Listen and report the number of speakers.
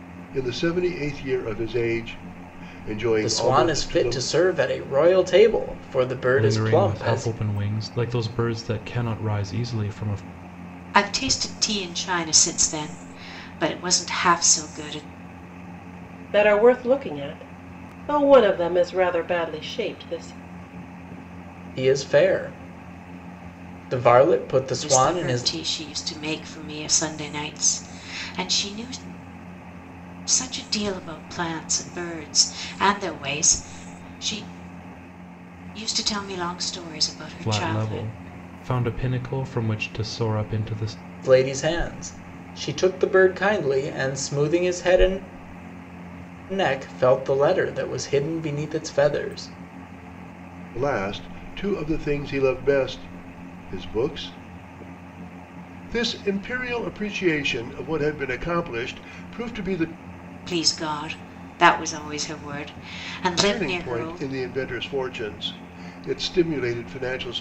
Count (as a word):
five